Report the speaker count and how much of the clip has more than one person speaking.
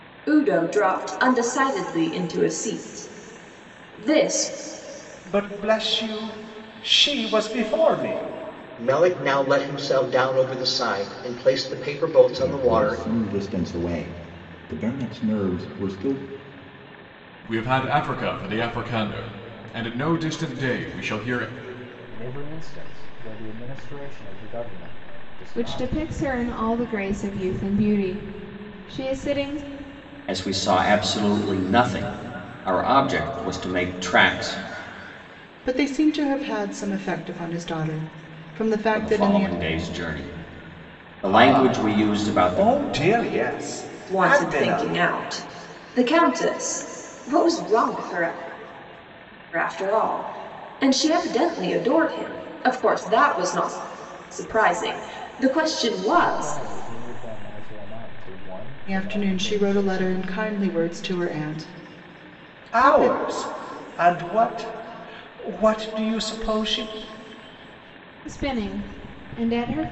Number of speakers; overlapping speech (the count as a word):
nine, about 9%